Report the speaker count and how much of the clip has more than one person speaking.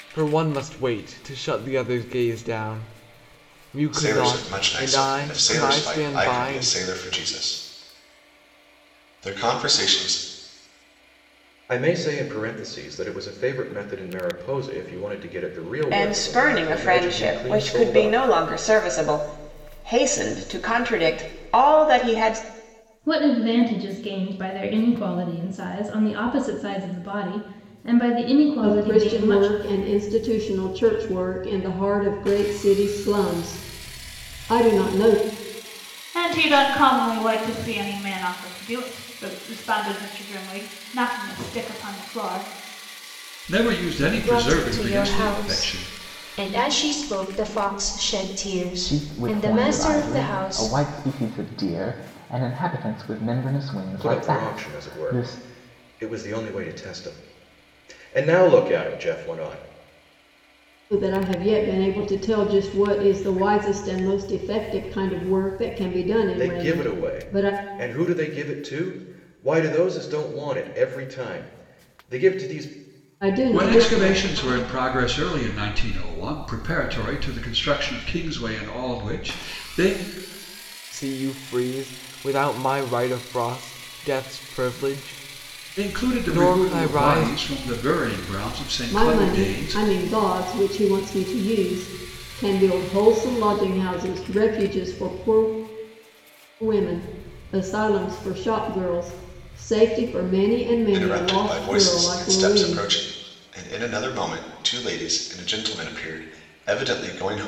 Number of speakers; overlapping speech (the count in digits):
10, about 17%